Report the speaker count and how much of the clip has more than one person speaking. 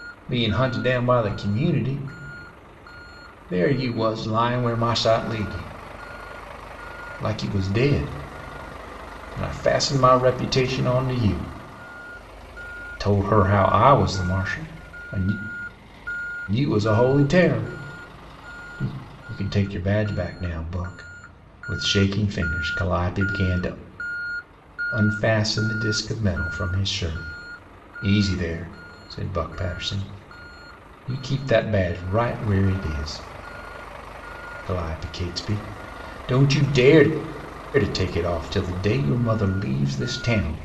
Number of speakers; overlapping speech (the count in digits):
1, no overlap